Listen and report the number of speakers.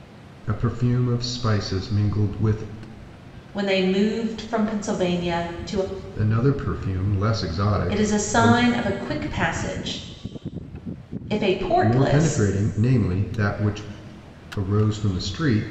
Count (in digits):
2